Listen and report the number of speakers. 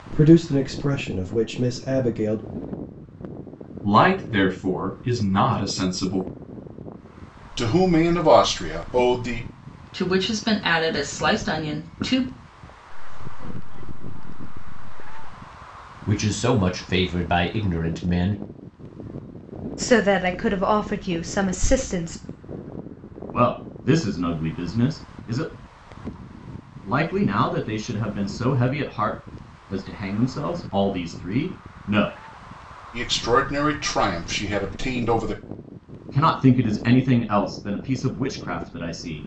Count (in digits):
8